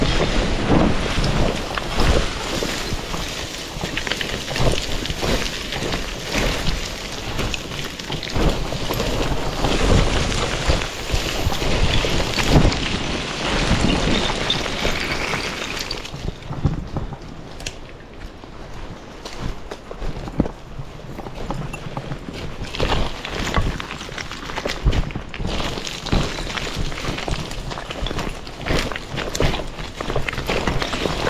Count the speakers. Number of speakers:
0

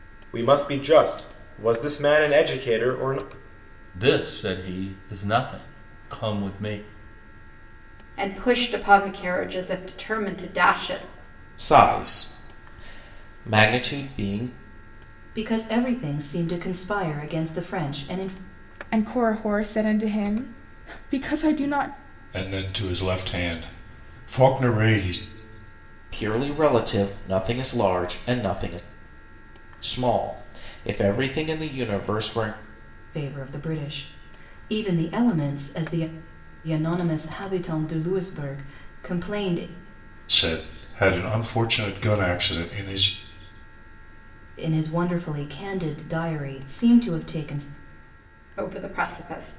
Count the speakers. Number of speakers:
7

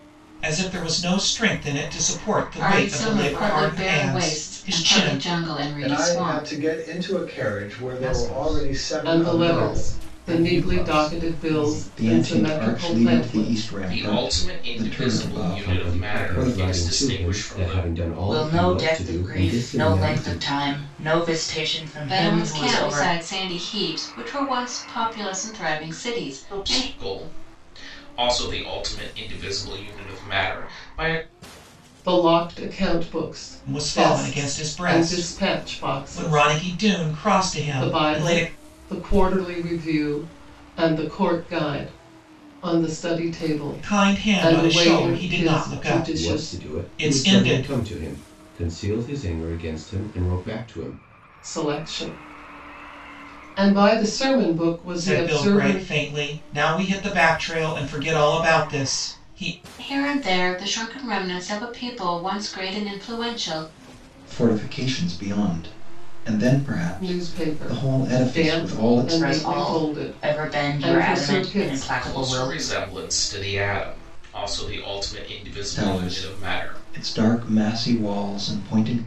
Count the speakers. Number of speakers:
9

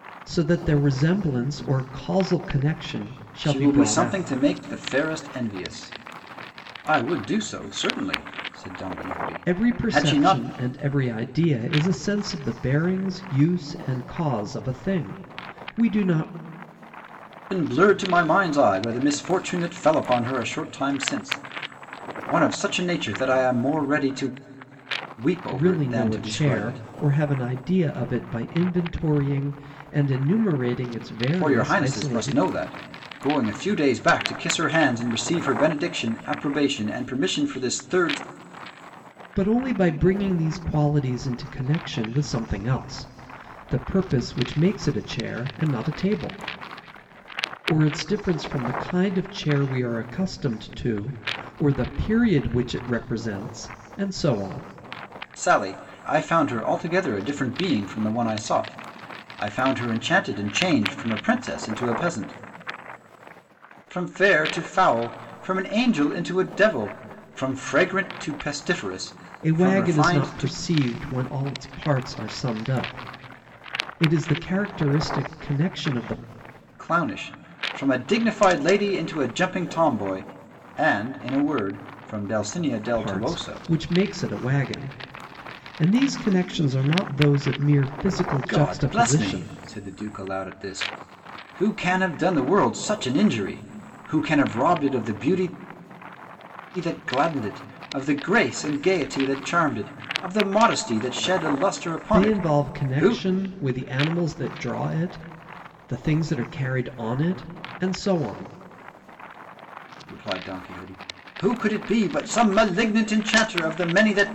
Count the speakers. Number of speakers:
2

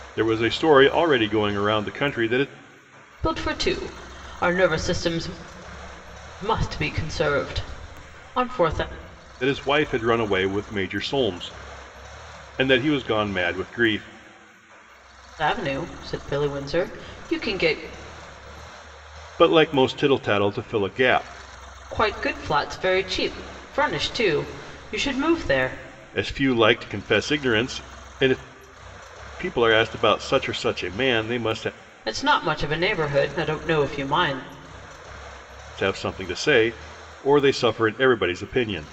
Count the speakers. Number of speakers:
2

